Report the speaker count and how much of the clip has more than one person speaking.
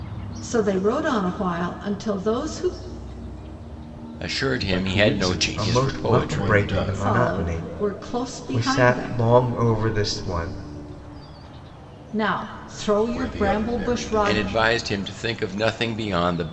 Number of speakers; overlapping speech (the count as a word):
four, about 33%